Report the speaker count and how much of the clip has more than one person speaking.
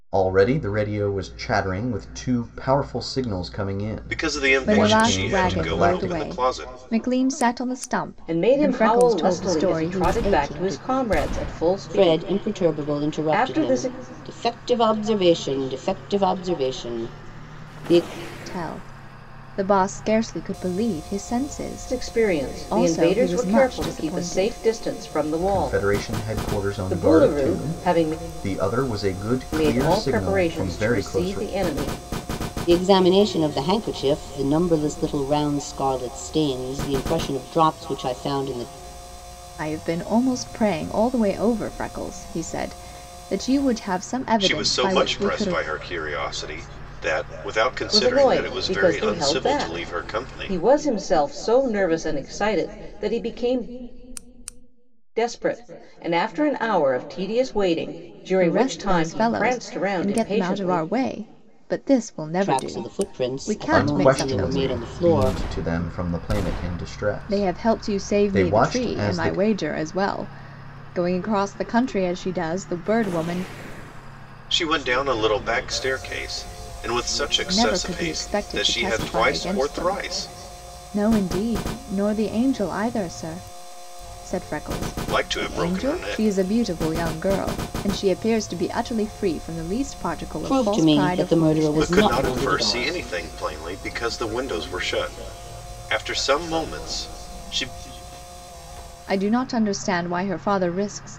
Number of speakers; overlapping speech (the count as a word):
five, about 33%